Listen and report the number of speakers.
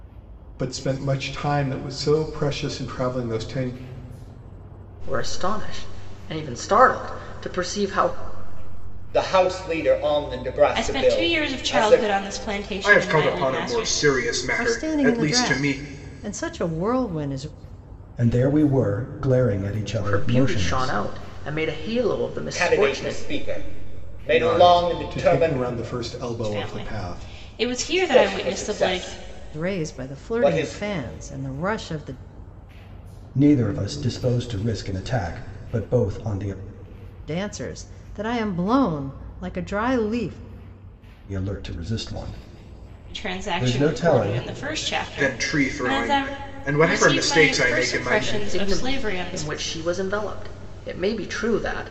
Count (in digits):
7